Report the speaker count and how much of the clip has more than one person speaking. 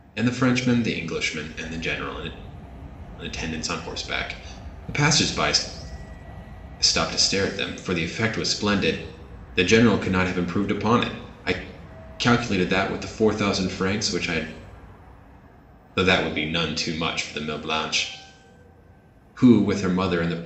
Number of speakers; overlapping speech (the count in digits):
1, no overlap